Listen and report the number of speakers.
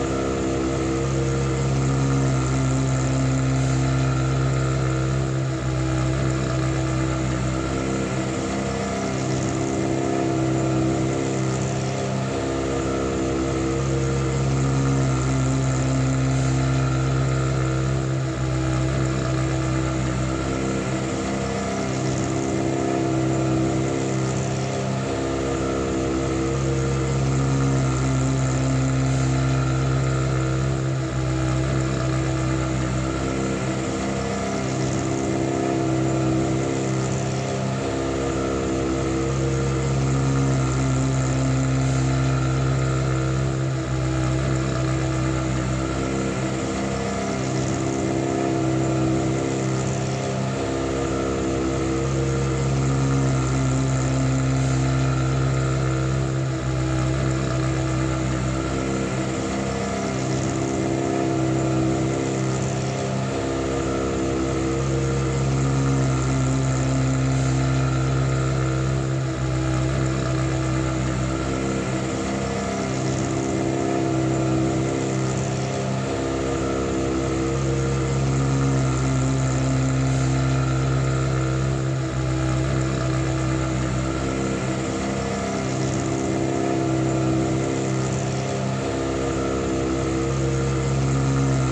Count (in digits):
0